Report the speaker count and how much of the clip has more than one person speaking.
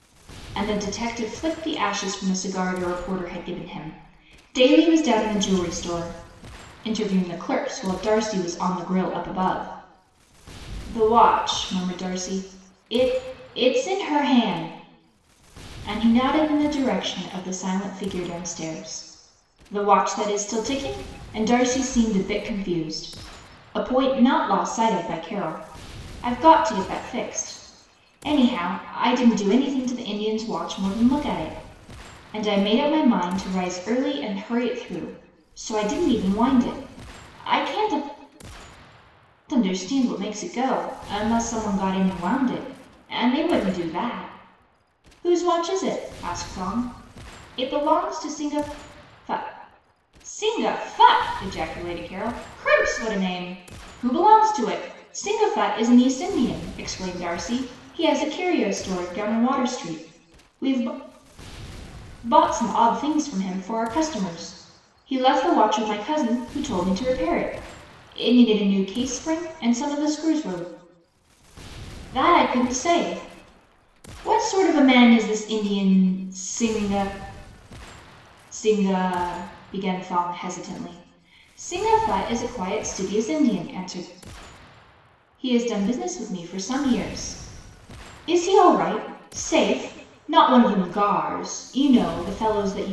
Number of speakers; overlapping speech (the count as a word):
one, no overlap